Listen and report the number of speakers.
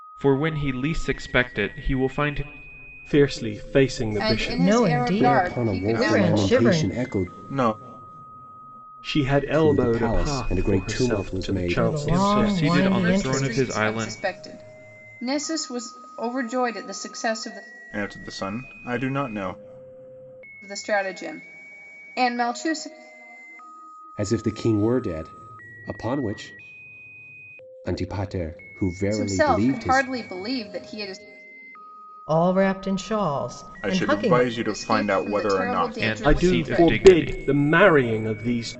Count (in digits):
6